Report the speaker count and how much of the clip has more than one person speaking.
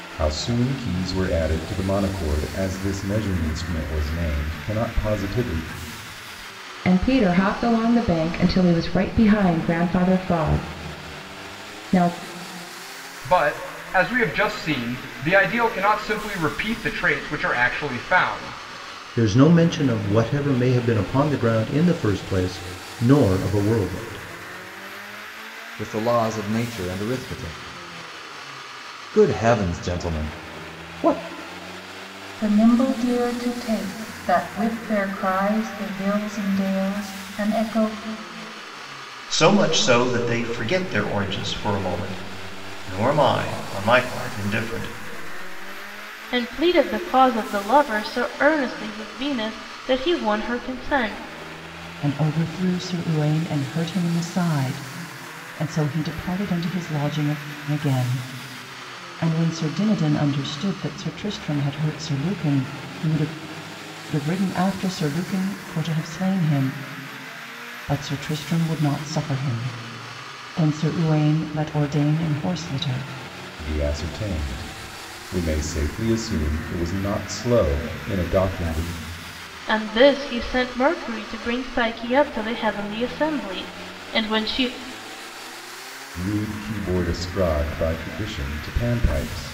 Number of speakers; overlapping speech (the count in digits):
9, no overlap